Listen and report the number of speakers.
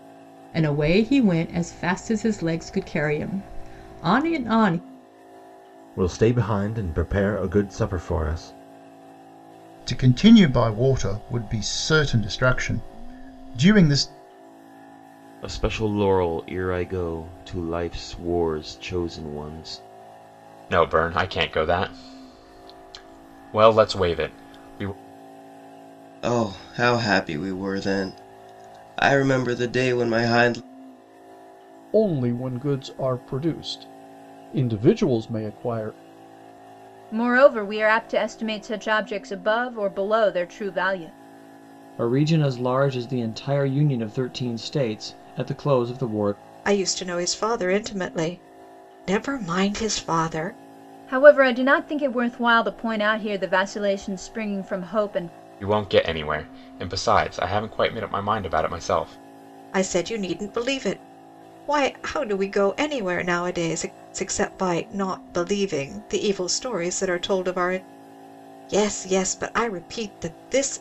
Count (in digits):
10